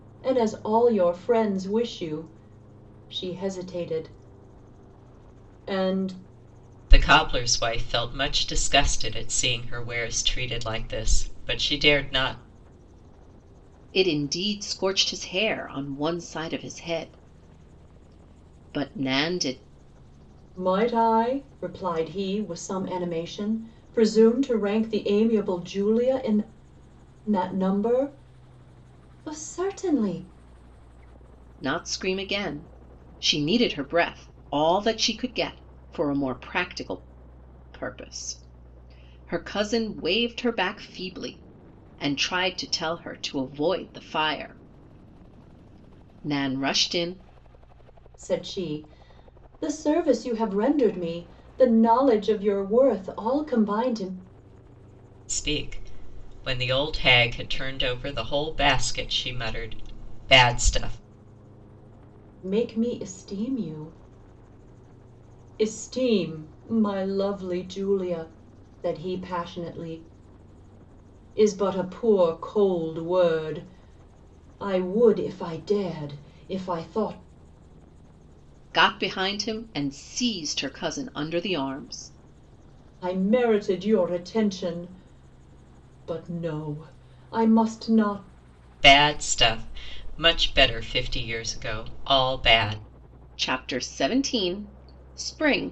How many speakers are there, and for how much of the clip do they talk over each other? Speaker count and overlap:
three, no overlap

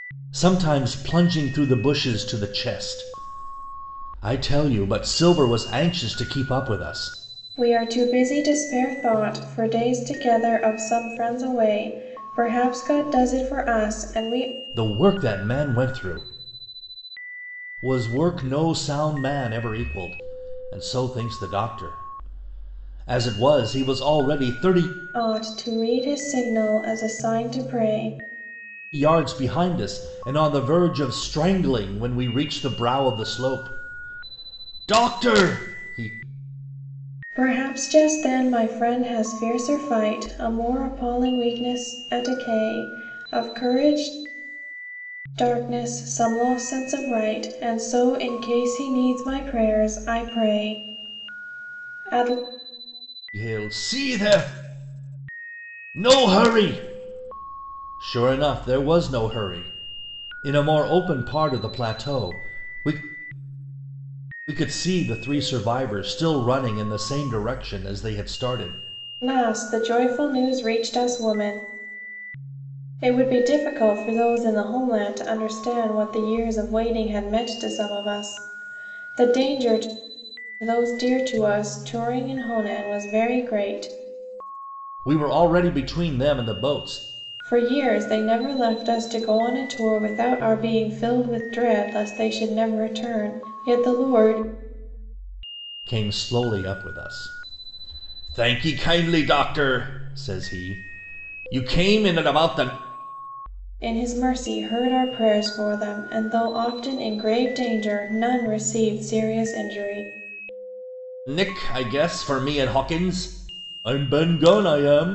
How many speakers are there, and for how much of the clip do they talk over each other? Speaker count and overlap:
two, no overlap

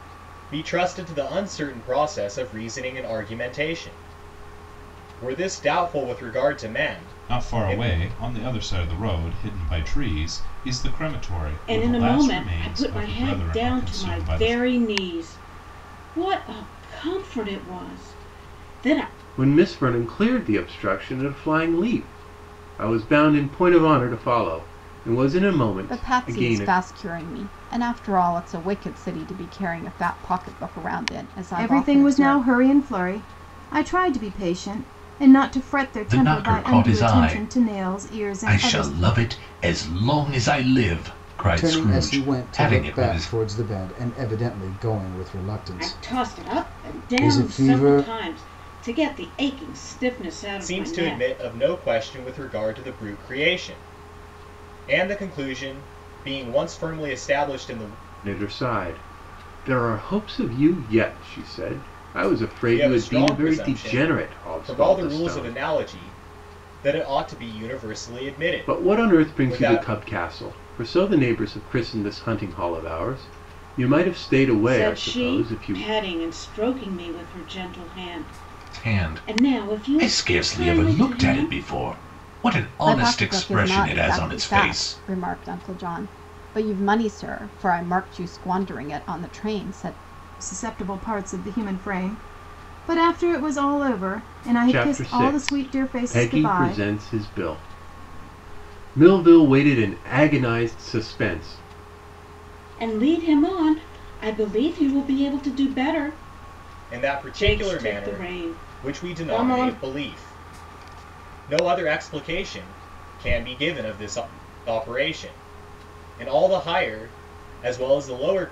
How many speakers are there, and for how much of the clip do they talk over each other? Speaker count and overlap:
eight, about 24%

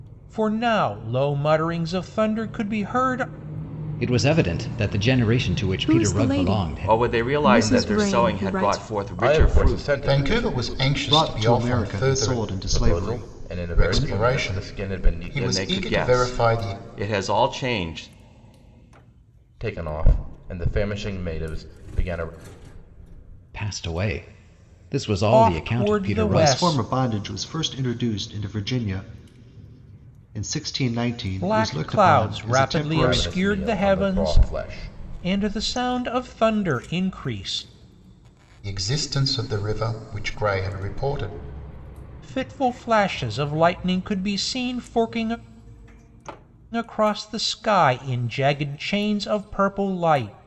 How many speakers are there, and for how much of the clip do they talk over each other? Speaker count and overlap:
seven, about 29%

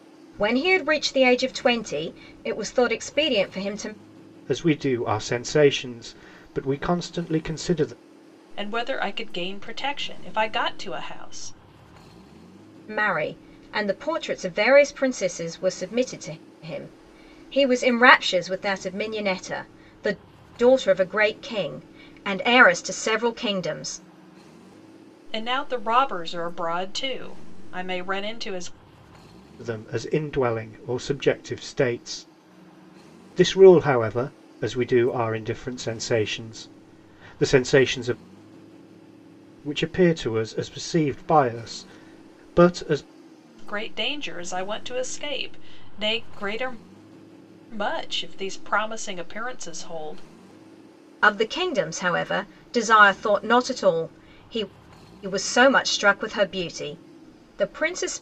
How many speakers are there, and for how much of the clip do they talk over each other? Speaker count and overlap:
three, no overlap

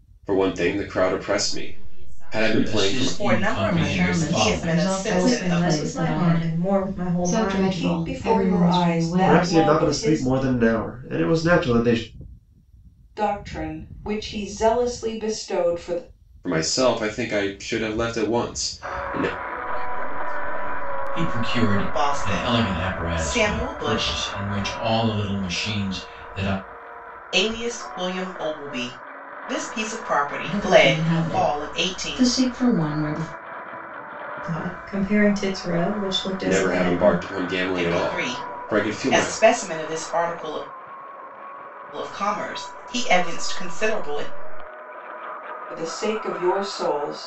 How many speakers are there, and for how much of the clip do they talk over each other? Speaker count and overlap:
nine, about 36%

